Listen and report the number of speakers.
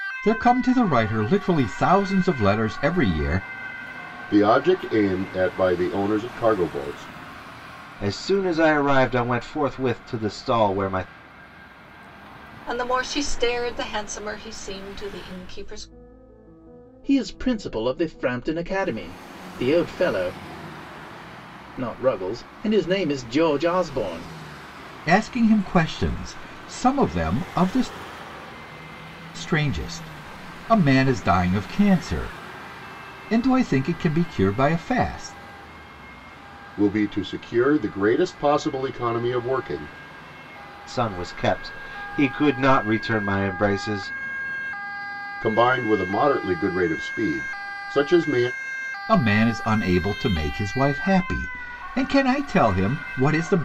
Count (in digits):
5